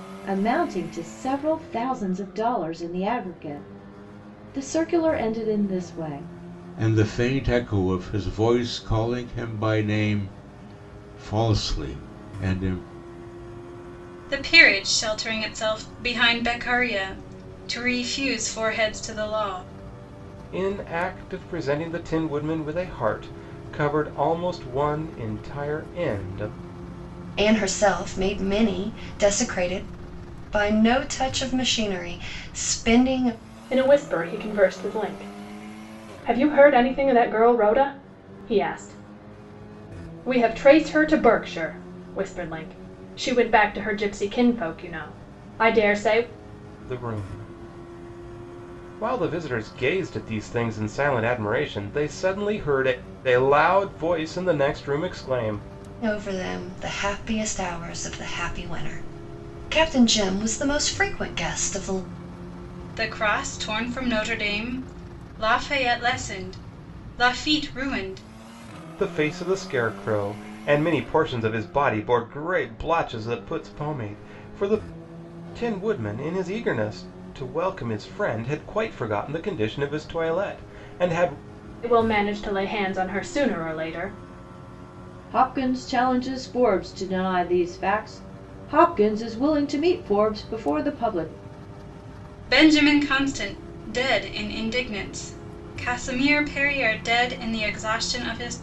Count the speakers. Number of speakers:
6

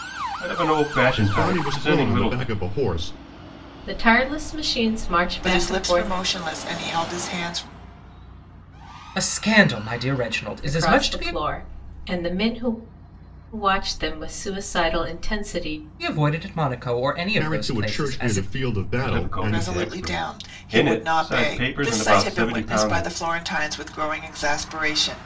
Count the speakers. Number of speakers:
5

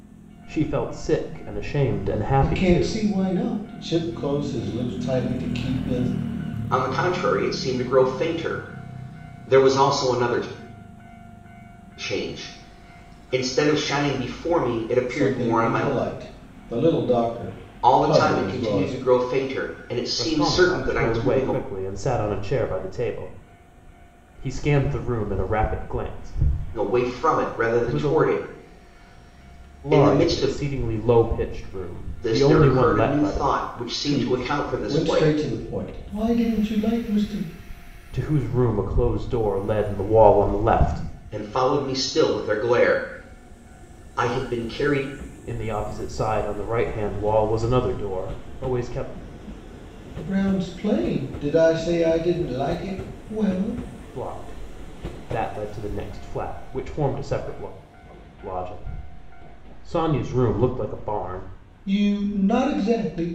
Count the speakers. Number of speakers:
3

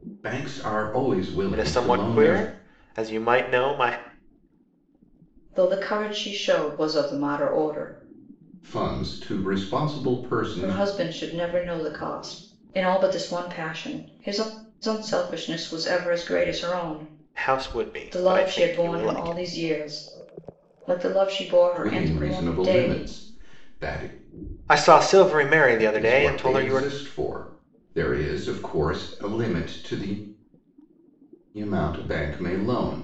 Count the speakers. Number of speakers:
3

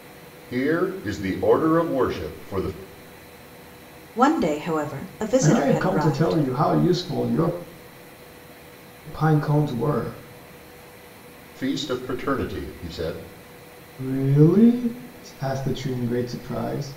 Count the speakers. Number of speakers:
3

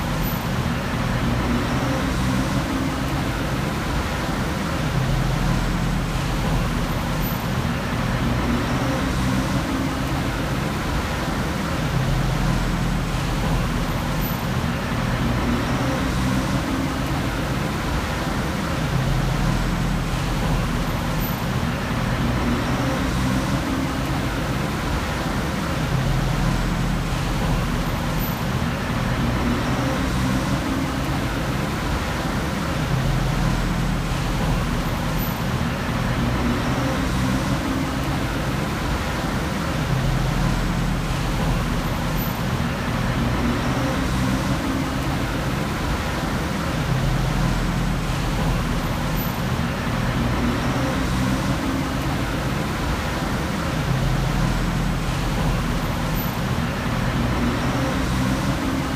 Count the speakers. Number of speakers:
0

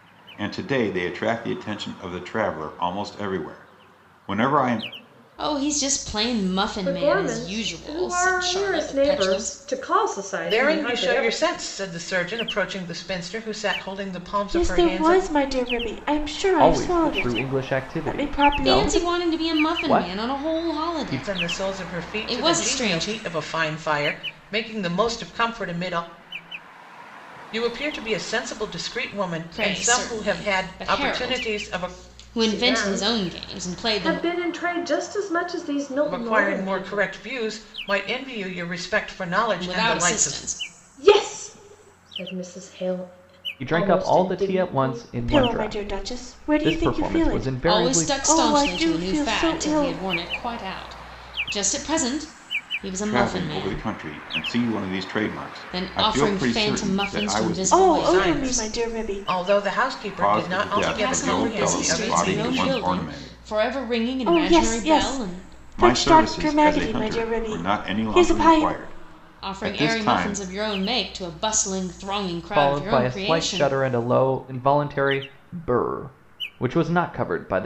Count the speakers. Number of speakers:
6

